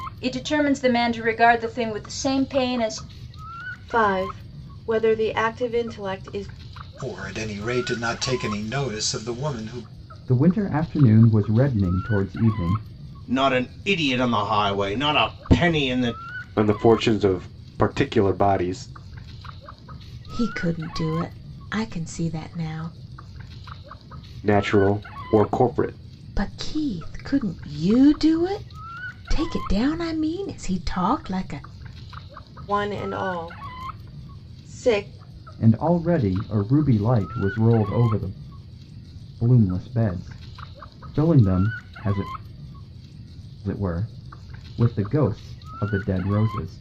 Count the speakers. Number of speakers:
7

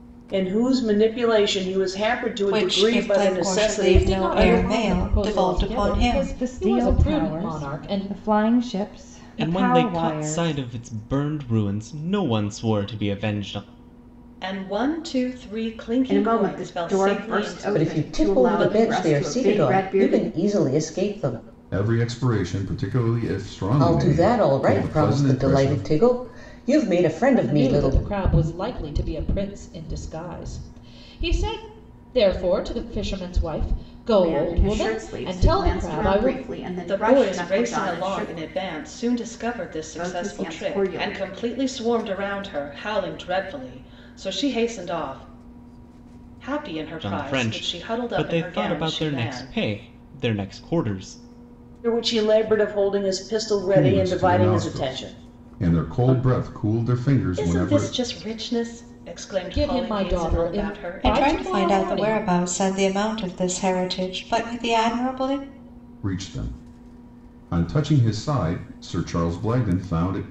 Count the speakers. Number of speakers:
9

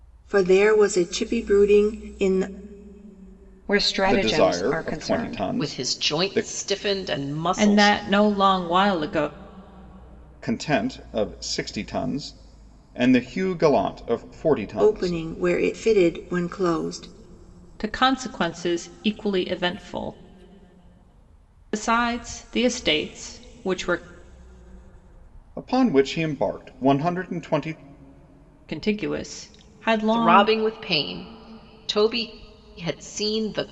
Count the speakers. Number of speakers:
5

